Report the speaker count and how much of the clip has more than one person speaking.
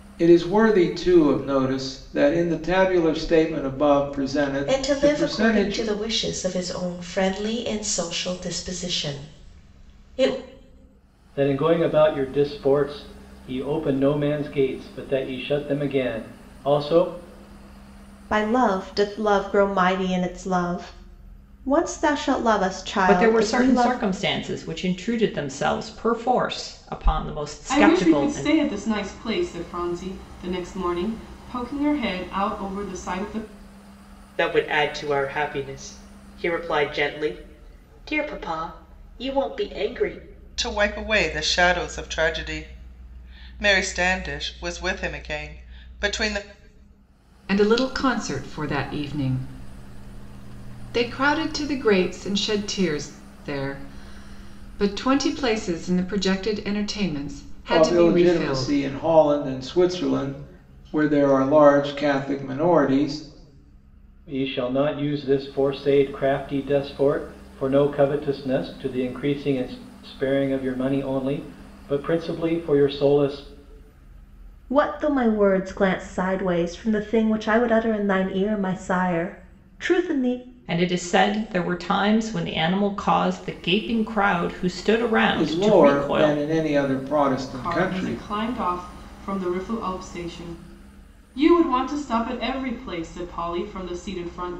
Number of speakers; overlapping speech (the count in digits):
9, about 6%